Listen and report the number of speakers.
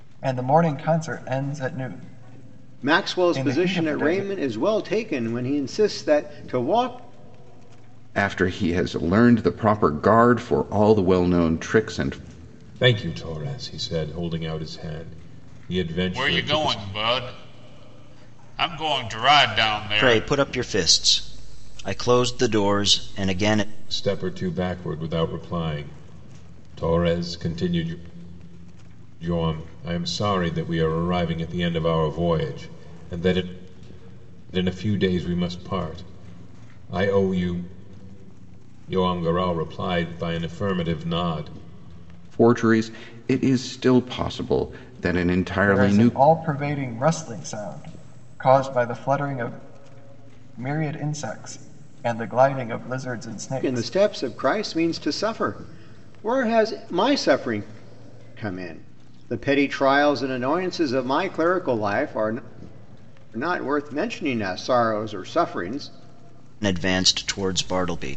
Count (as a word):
six